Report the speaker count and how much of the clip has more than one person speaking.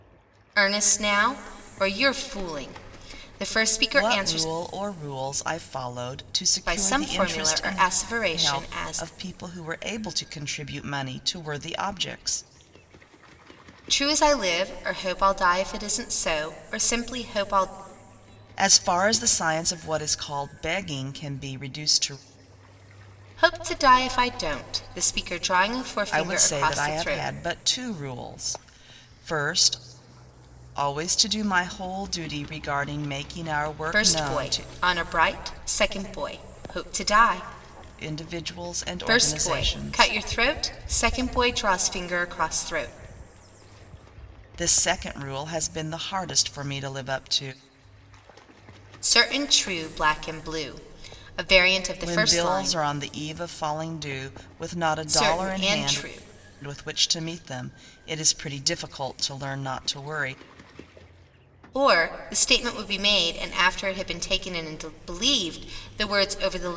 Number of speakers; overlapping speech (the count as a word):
two, about 12%